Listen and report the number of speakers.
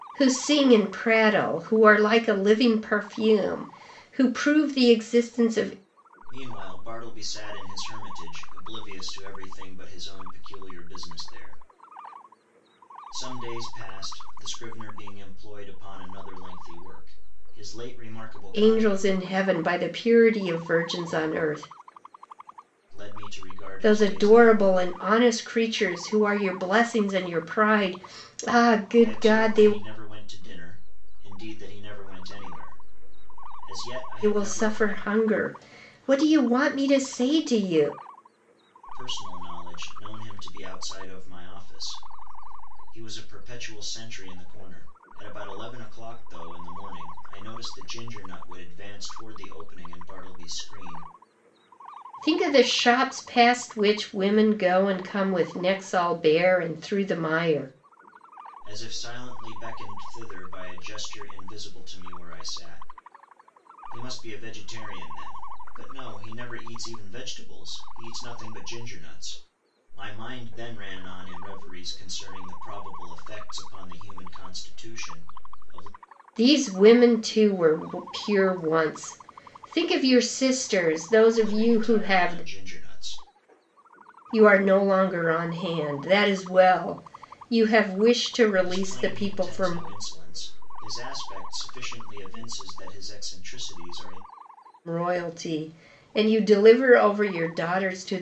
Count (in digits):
2